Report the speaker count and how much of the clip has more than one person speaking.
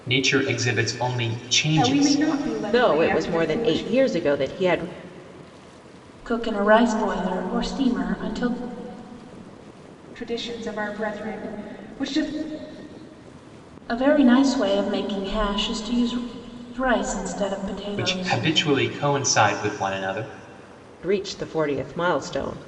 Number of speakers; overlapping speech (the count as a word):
four, about 10%